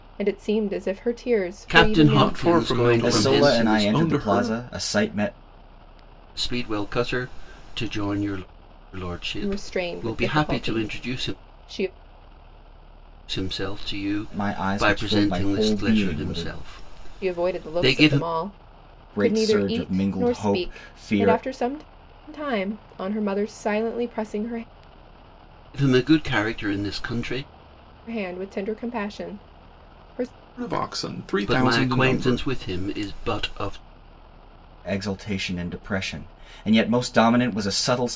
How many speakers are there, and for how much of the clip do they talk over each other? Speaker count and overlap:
4, about 30%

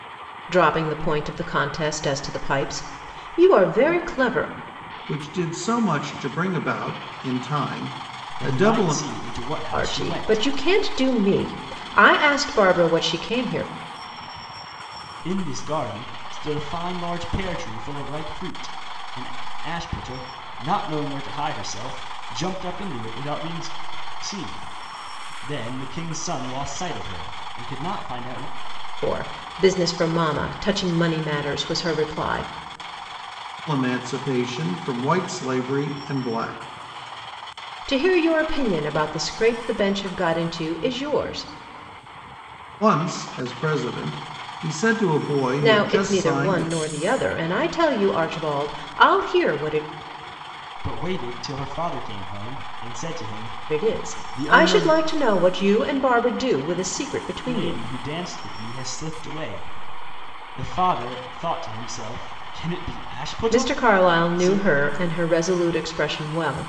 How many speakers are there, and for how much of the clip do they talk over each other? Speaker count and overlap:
3, about 8%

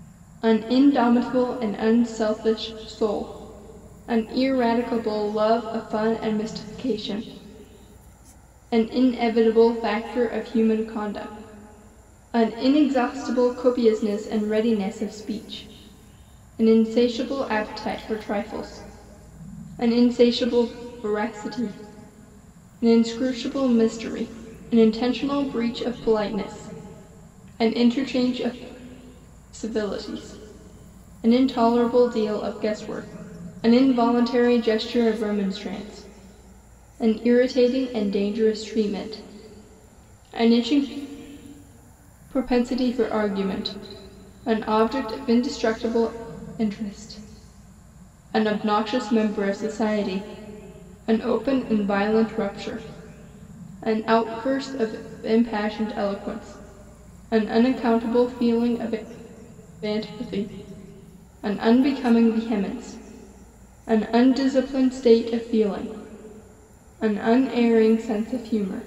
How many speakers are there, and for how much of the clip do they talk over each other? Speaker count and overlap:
1, no overlap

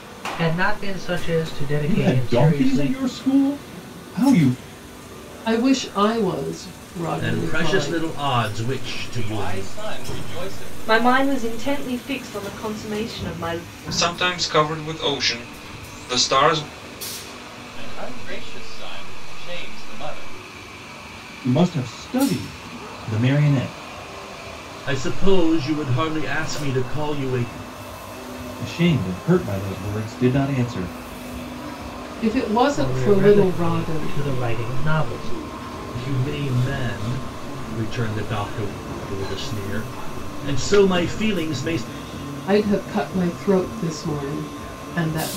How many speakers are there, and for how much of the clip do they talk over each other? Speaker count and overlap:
7, about 11%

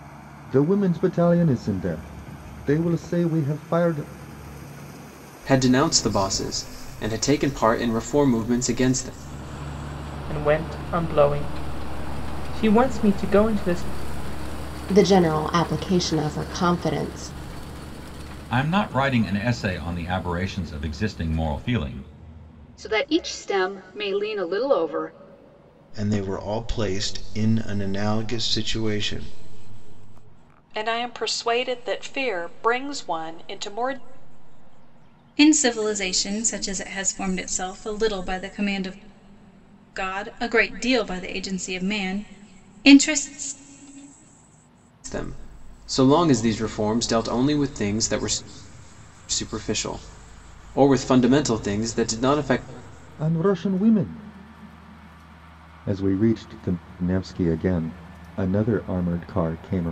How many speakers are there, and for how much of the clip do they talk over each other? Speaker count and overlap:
9, no overlap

